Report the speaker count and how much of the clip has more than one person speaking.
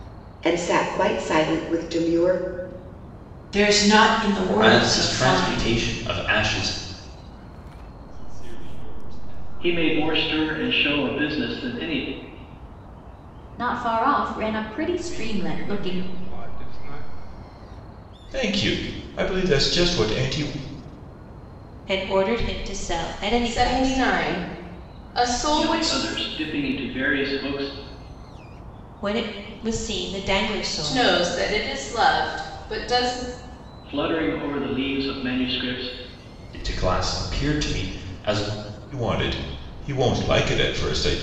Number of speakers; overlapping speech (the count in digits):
10, about 11%